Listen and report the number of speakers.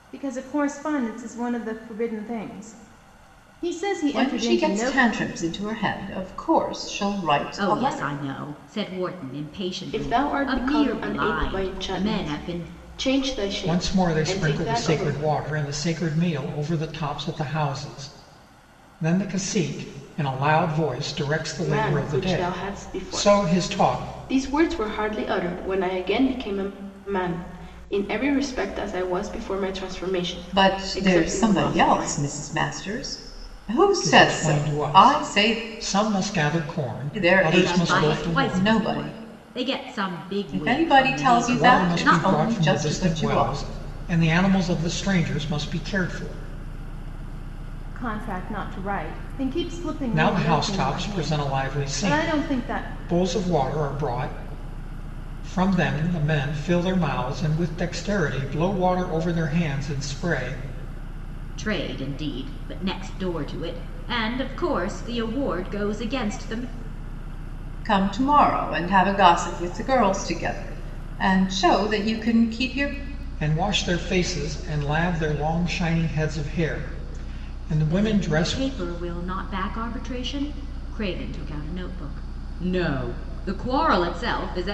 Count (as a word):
five